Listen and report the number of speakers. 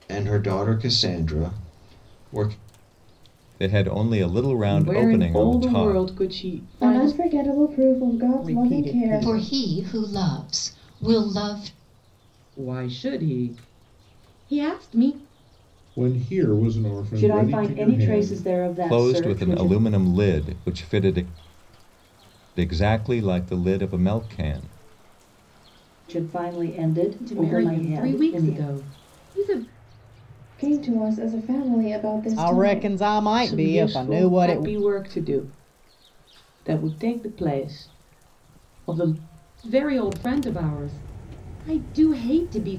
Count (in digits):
9